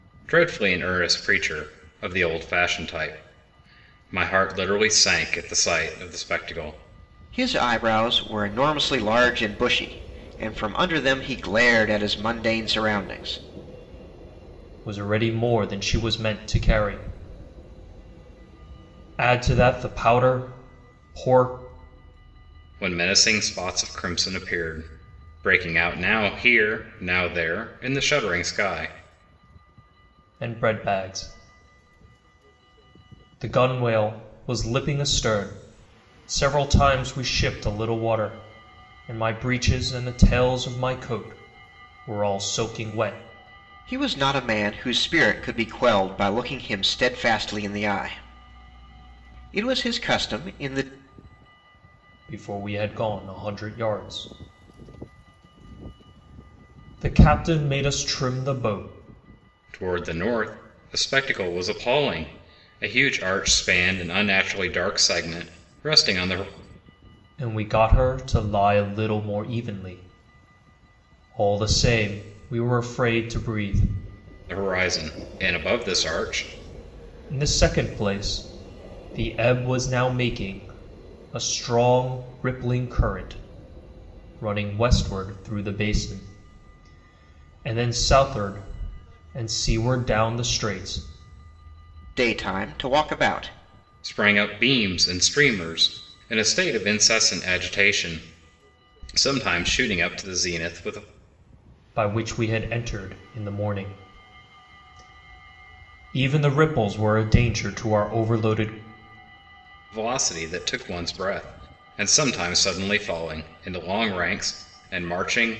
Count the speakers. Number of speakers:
3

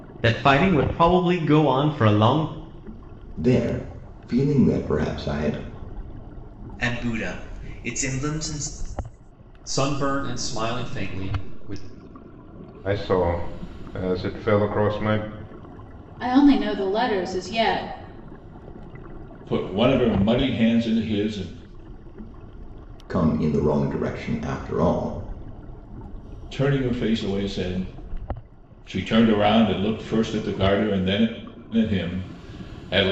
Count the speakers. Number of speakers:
7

